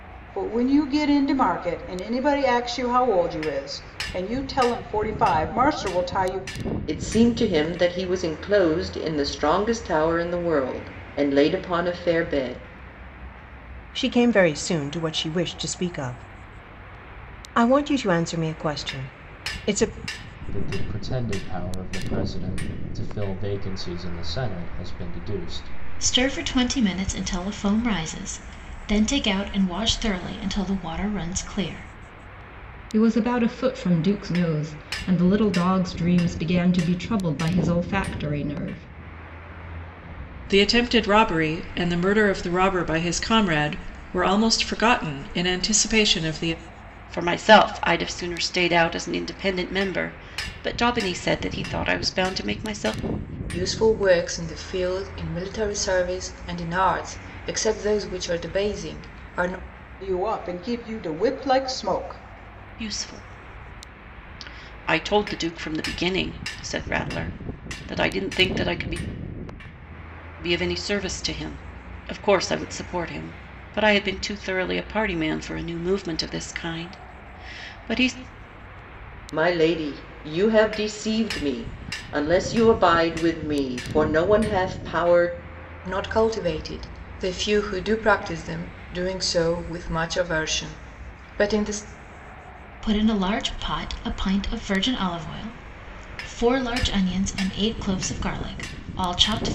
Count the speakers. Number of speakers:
nine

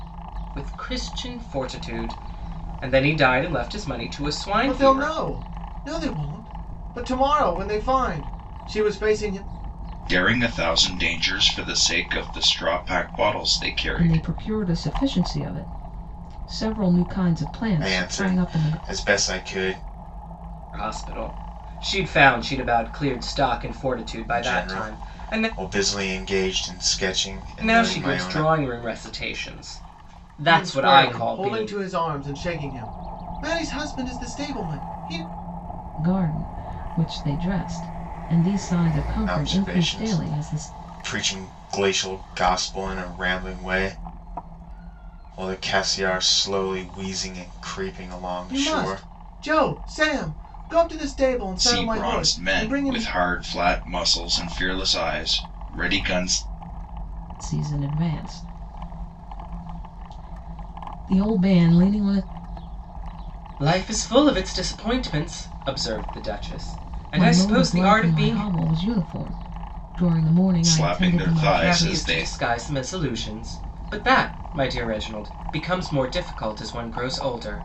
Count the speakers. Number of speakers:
five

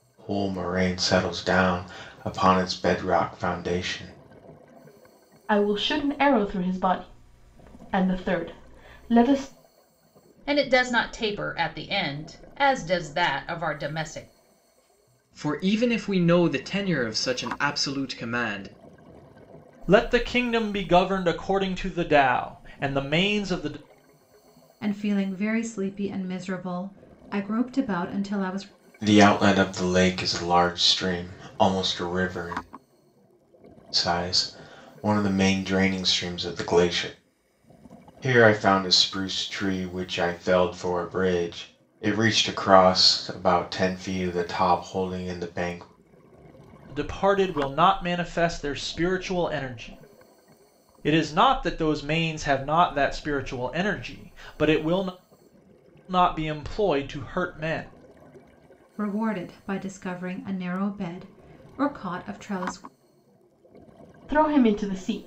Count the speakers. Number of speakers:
six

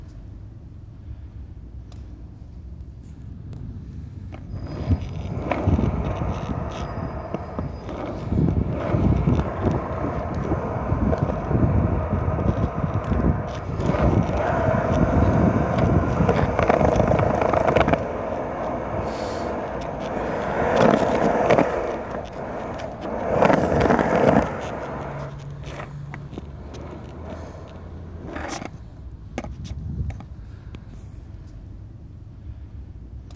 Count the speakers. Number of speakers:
zero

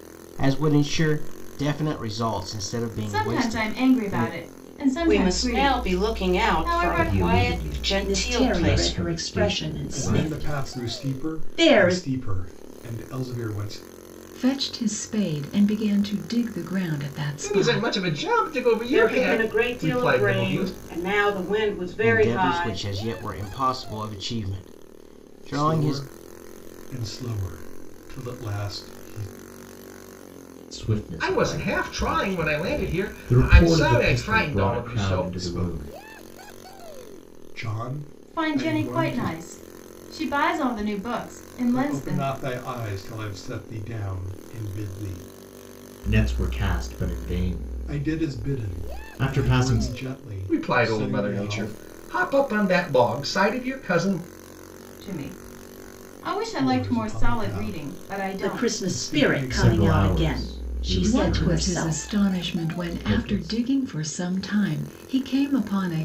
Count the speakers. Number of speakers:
eight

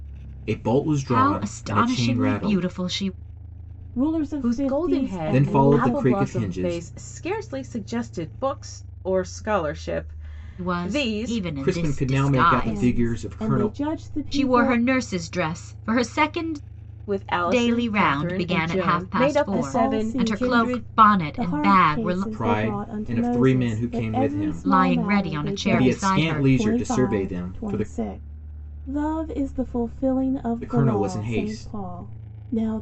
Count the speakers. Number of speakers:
four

